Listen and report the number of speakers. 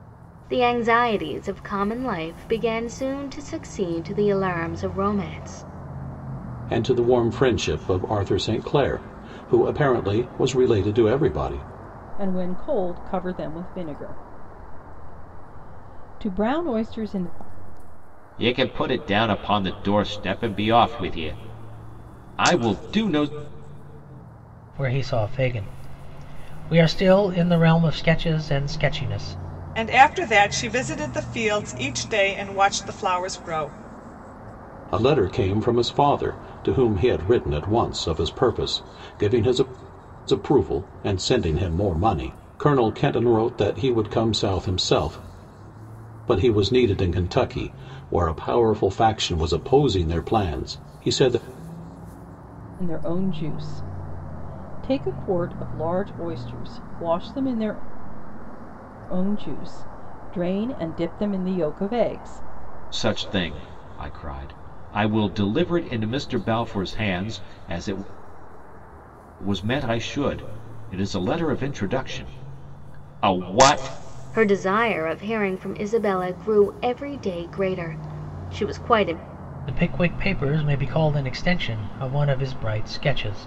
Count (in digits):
6